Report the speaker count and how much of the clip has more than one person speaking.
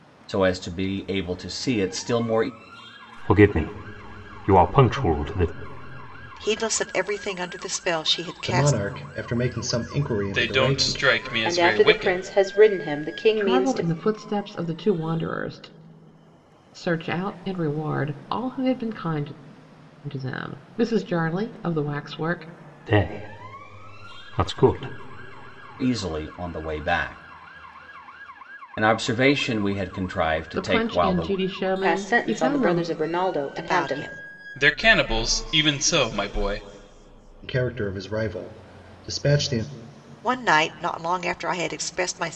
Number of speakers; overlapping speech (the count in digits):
7, about 12%